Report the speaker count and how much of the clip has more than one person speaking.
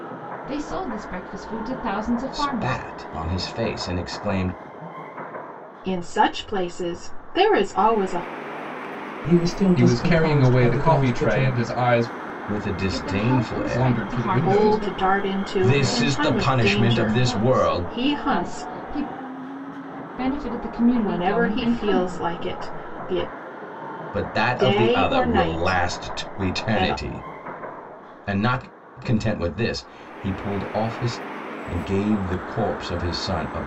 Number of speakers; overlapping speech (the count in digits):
5, about 36%